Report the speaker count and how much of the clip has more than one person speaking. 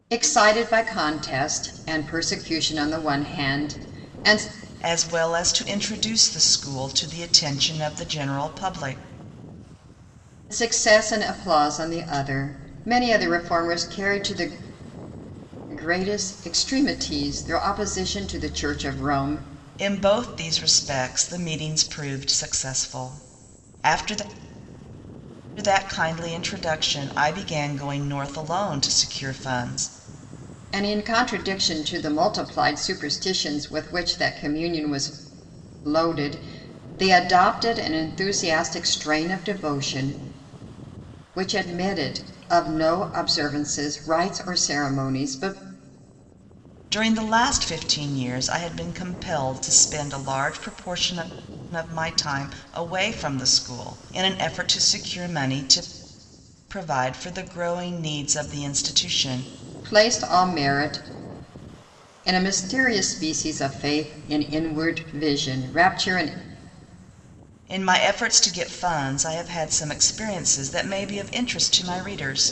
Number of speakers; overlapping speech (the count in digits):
2, no overlap